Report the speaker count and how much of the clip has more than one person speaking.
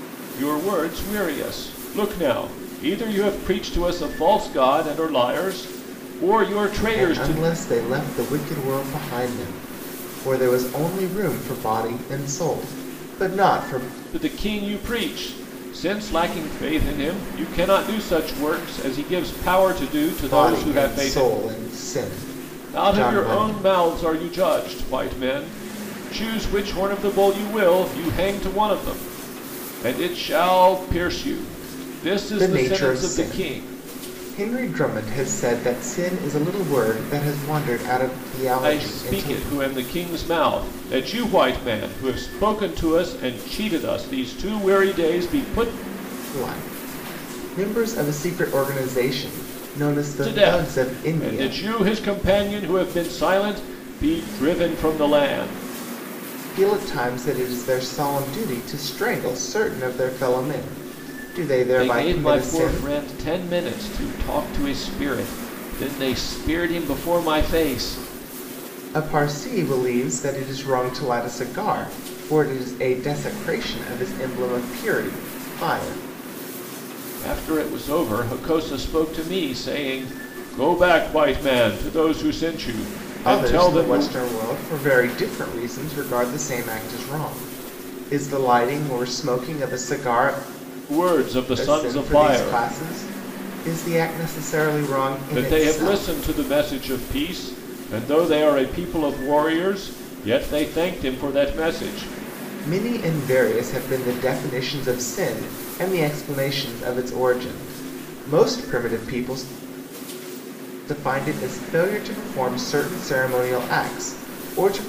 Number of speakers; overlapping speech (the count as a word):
two, about 9%